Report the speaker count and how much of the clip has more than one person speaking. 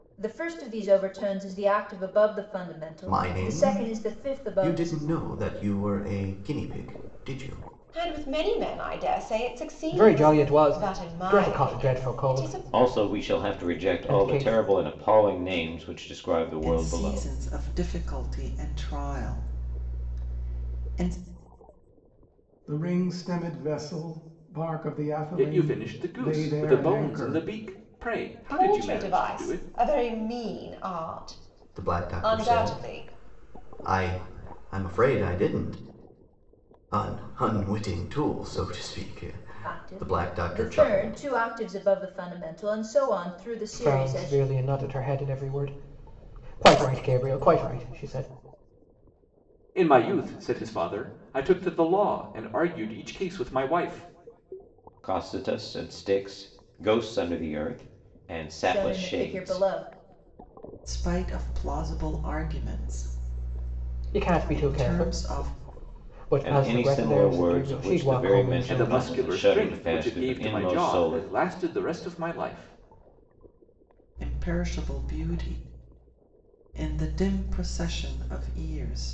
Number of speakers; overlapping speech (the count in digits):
8, about 28%